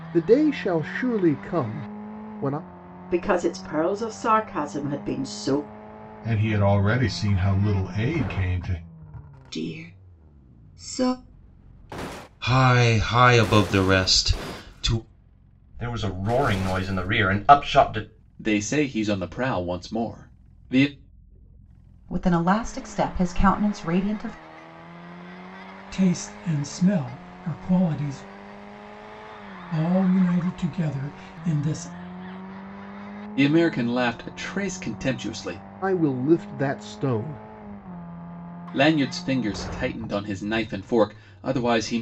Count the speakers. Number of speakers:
9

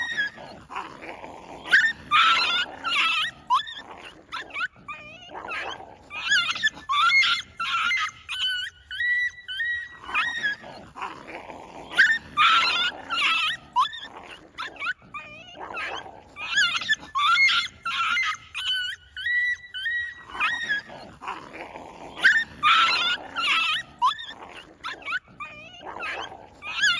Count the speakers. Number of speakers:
0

